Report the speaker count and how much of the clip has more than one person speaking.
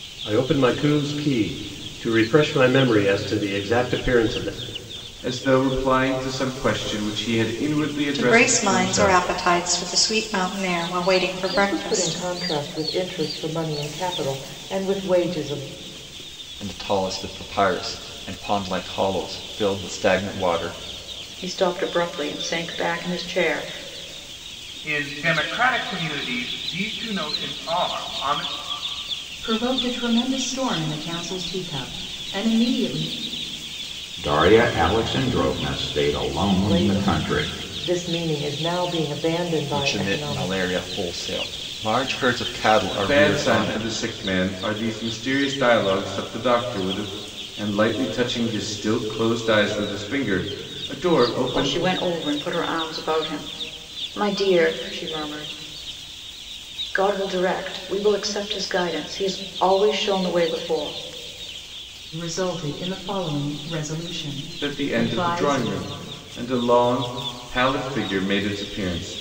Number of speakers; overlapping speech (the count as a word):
nine, about 9%